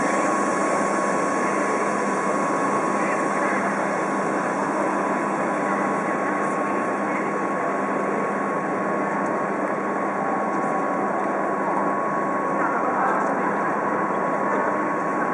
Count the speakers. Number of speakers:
zero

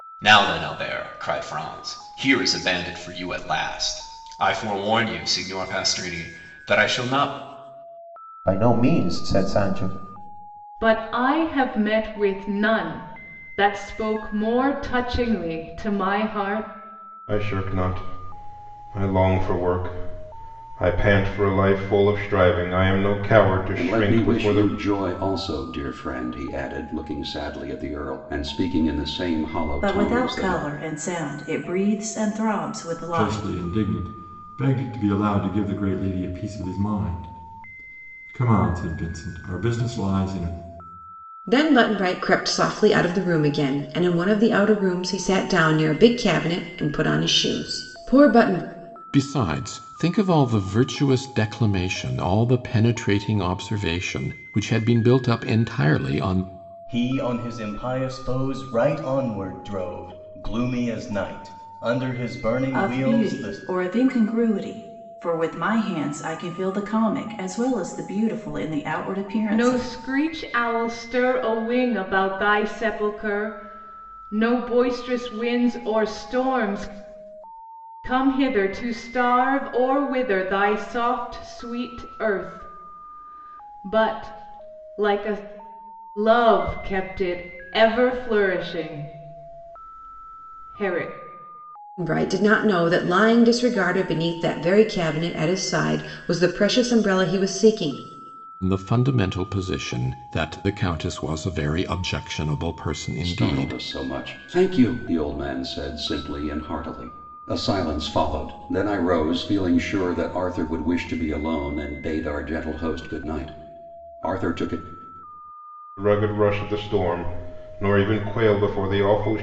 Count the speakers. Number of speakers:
ten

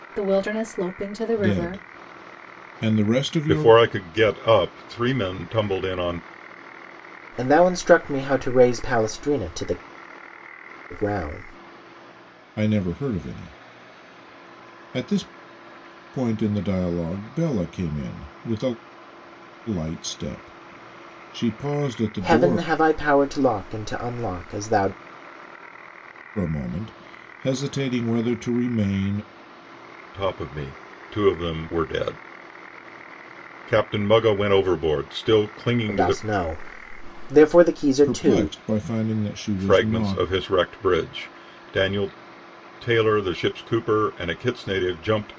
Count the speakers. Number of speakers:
four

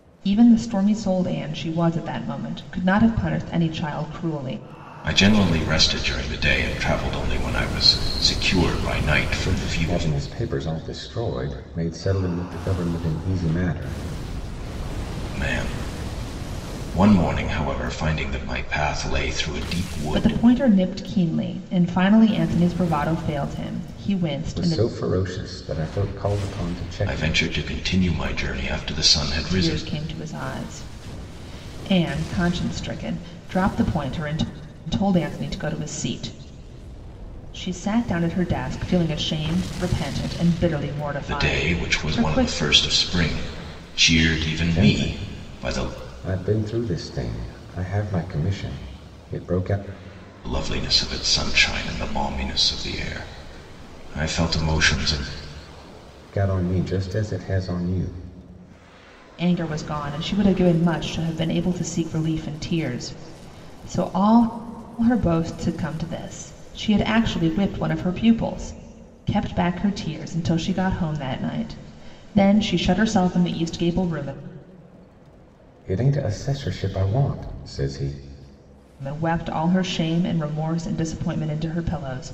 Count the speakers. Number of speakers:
three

